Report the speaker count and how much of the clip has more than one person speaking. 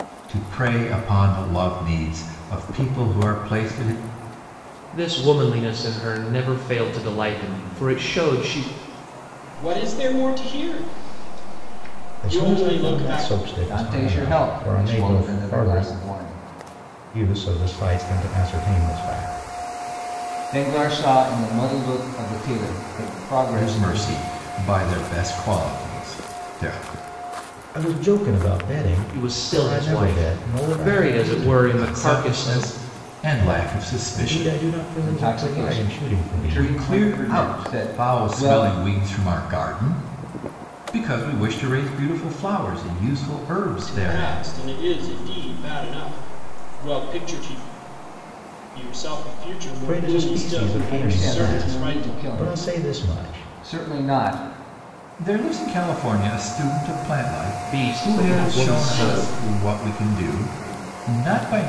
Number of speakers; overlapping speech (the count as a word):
five, about 30%